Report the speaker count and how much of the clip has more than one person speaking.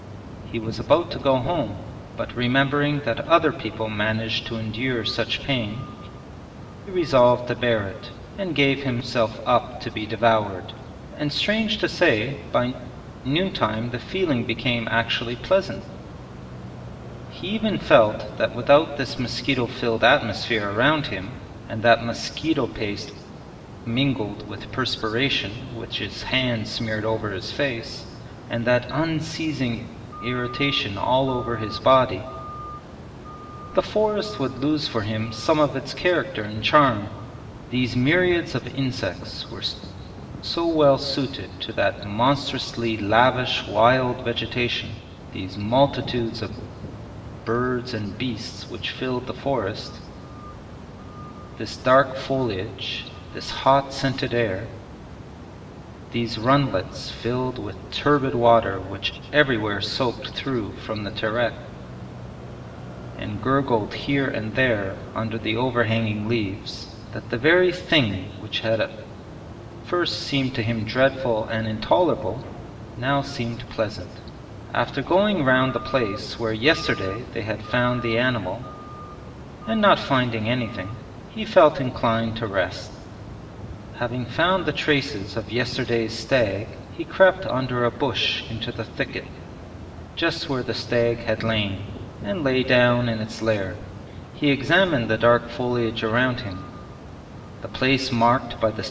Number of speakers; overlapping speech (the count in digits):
1, no overlap